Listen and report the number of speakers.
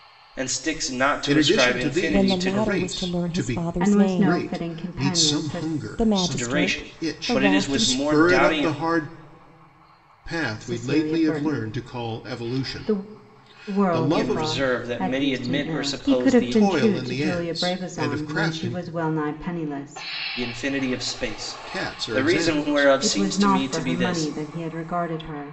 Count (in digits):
4